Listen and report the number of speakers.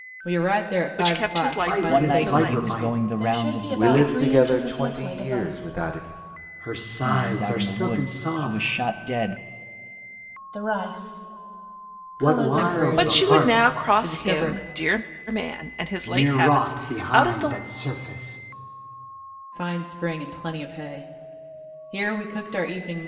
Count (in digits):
6